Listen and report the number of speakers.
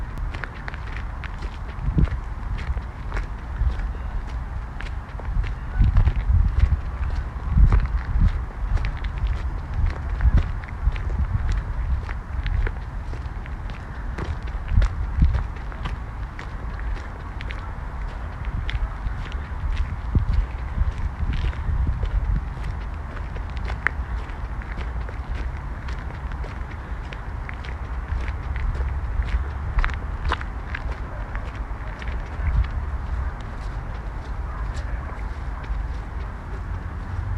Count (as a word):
zero